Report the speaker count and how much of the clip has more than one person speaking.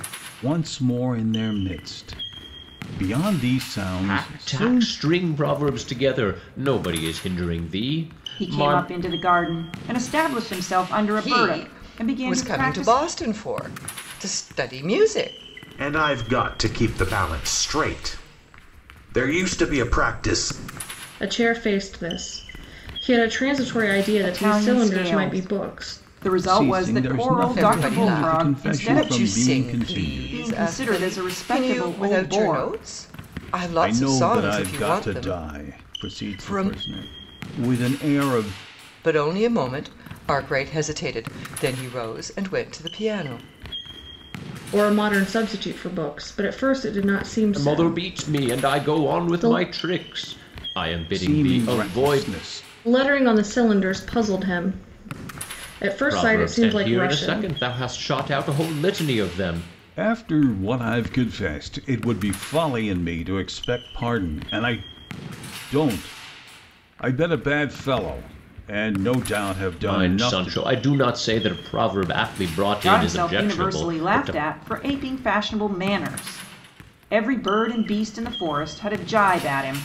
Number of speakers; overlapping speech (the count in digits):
6, about 27%